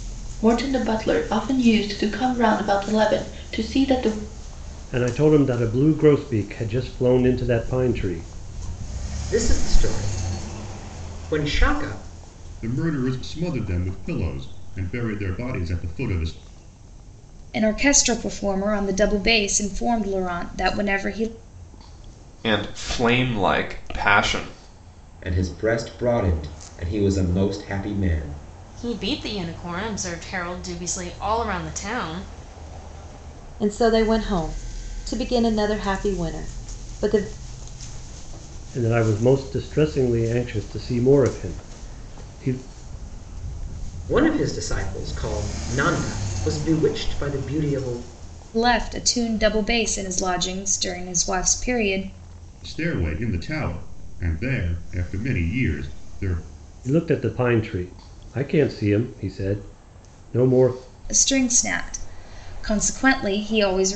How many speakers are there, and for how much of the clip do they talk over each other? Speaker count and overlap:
nine, no overlap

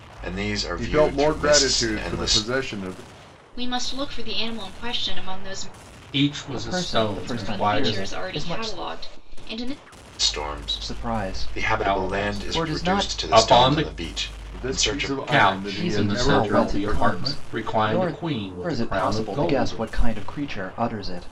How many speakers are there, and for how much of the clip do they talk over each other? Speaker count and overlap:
five, about 55%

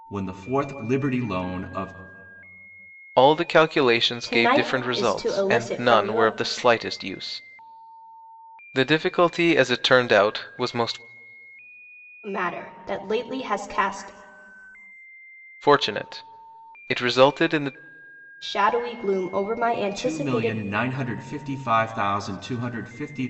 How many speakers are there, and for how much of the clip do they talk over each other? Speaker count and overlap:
three, about 12%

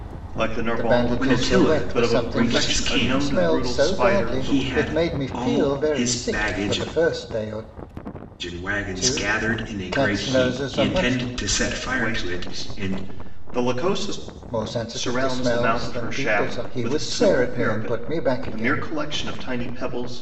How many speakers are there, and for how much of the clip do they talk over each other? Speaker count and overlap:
three, about 67%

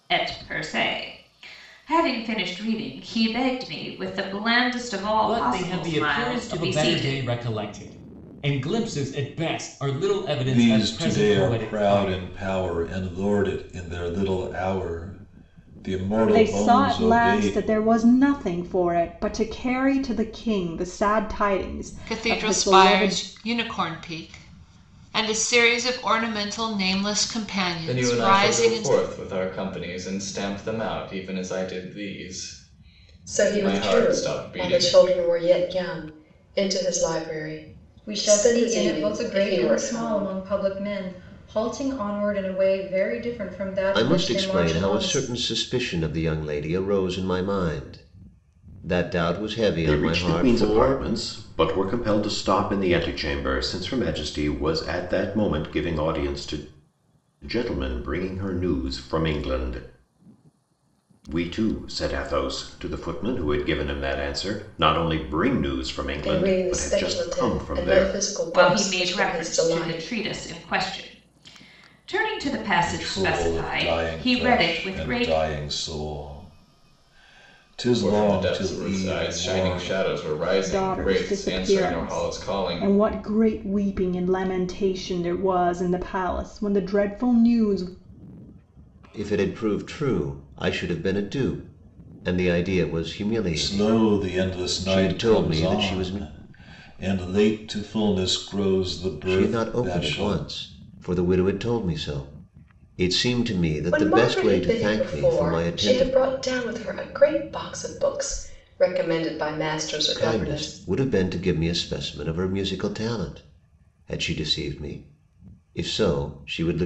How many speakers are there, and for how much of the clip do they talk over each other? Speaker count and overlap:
ten, about 27%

